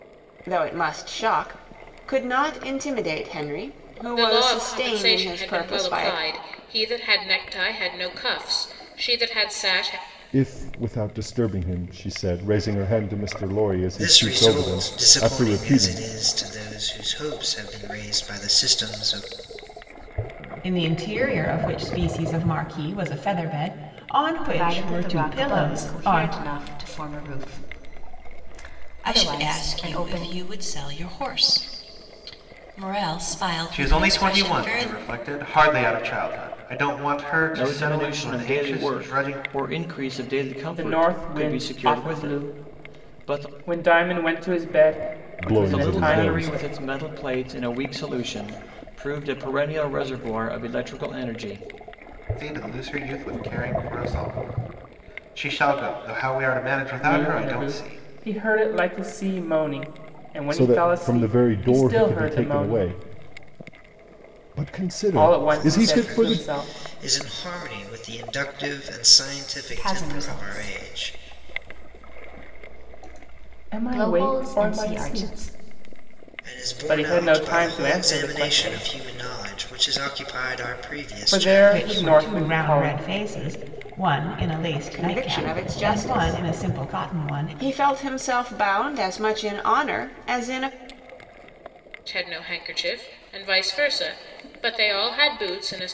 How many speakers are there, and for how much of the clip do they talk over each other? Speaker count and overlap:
ten, about 32%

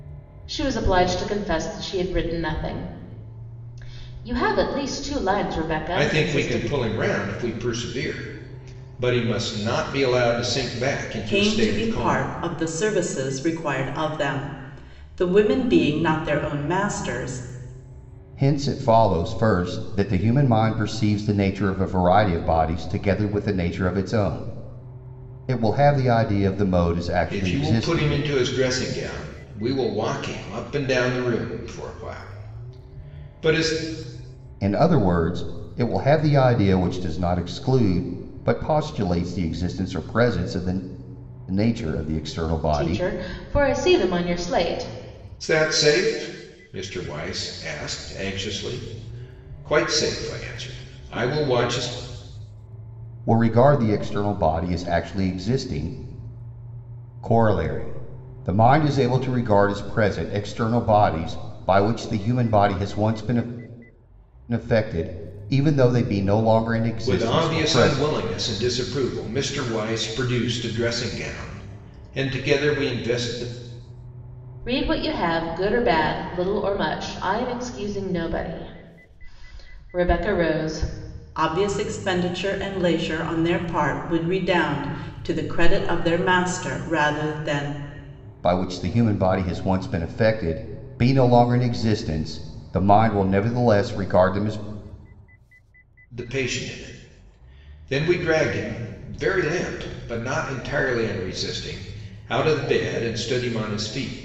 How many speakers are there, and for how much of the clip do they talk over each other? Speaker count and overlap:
four, about 4%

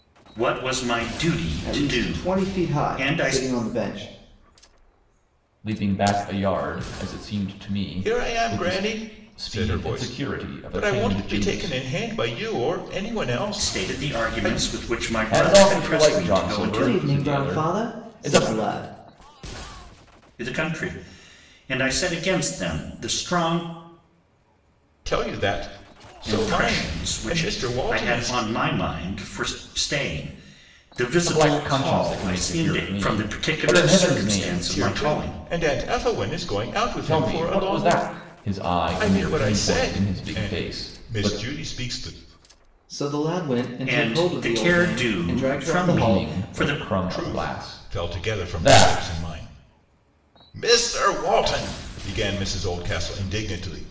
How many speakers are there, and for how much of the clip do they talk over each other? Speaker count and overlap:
four, about 45%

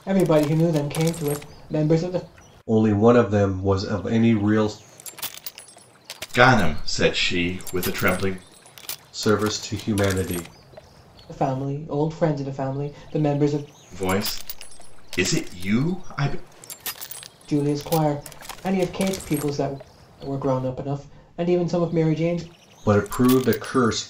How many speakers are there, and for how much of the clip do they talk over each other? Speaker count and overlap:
three, no overlap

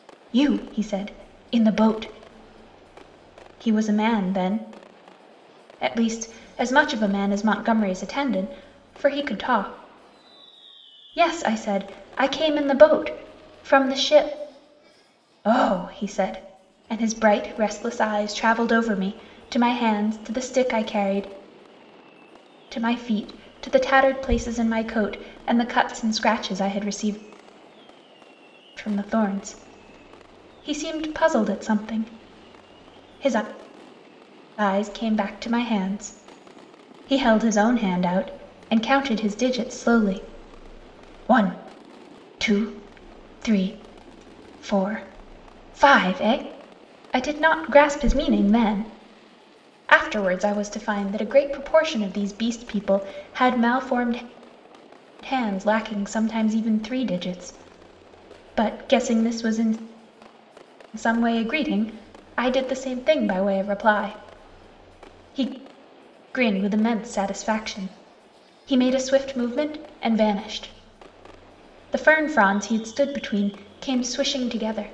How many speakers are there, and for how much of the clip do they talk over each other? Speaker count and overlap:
one, no overlap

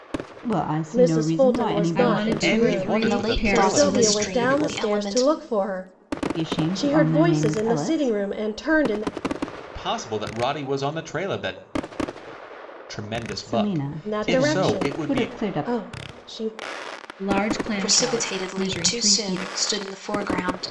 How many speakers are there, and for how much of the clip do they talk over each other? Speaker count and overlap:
five, about 48%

